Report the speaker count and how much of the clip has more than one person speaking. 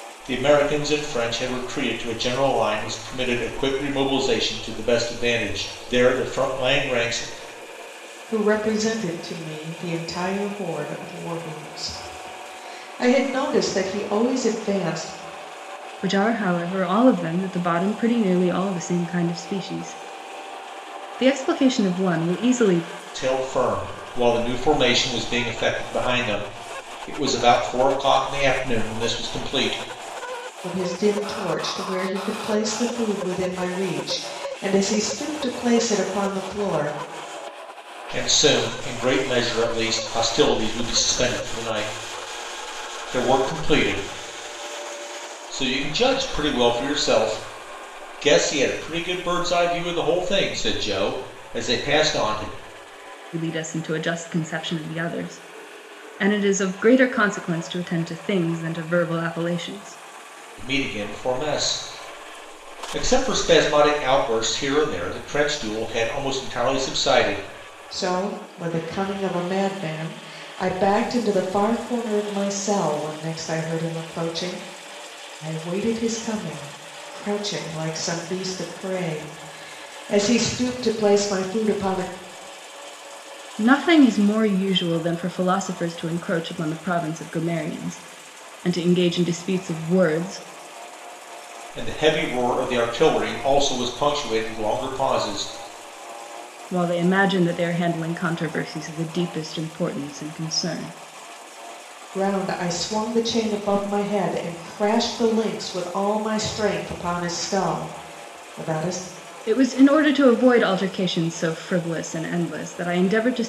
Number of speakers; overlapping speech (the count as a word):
three, no overlap